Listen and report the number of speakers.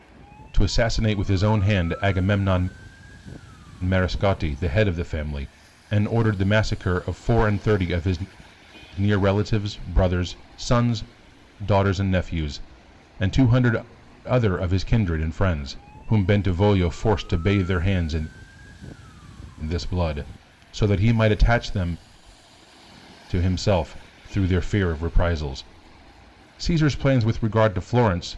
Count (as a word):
one